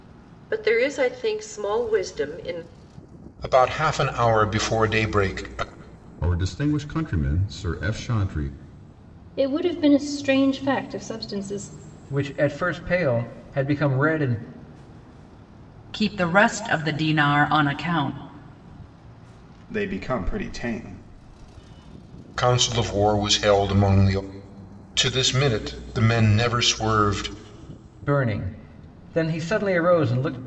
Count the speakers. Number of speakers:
7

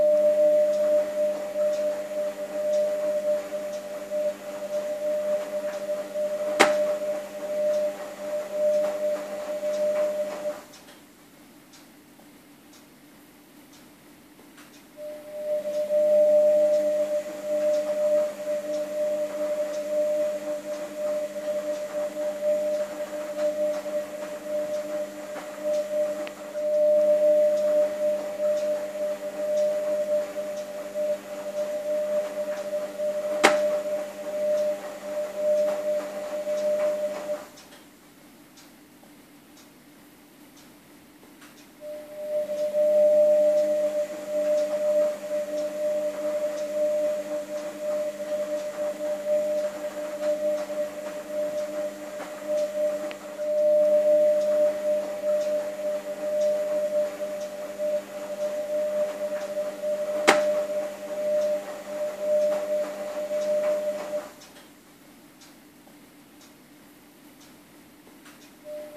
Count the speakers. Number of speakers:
0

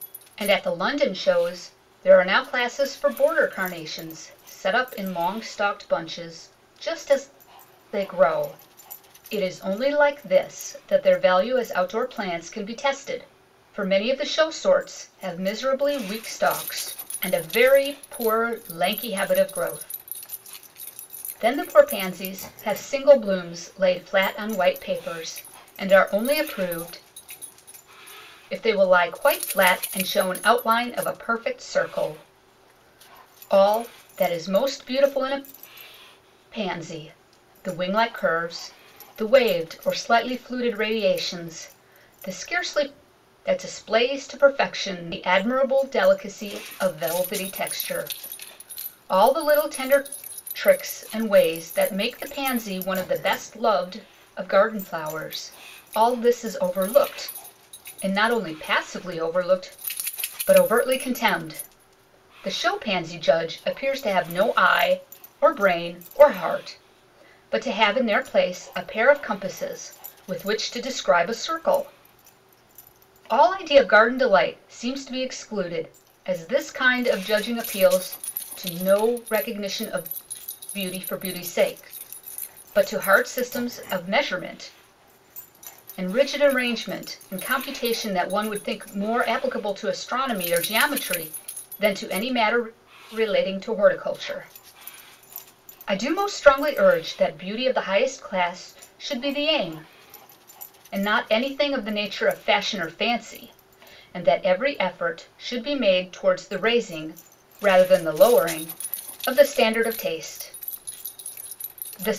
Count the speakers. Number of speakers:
1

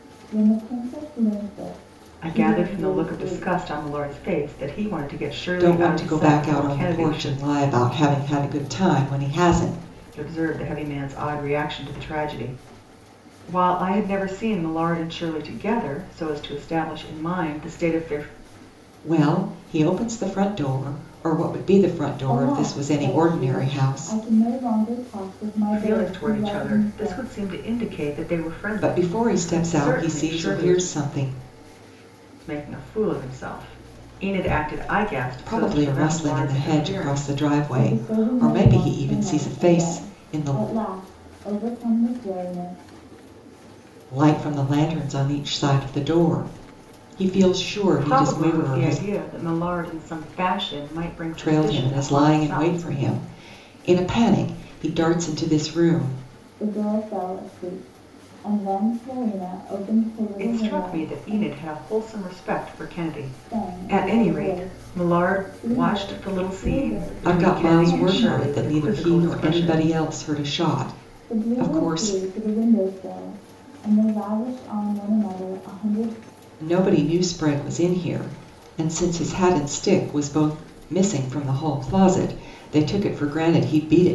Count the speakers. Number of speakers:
3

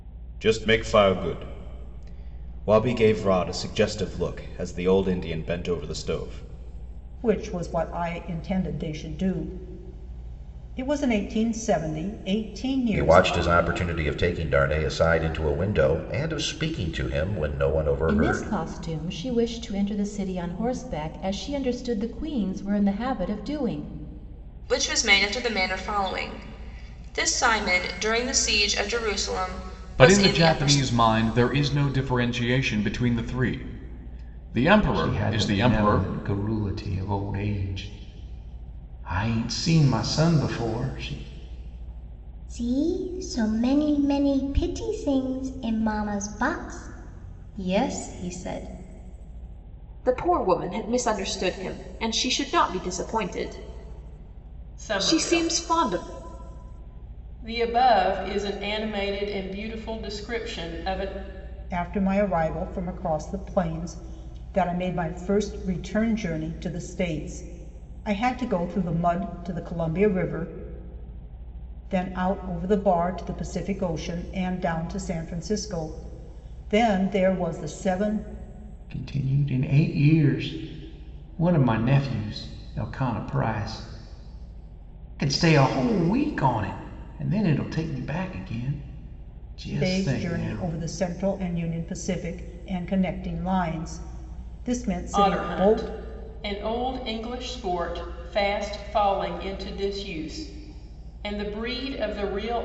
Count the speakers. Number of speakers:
10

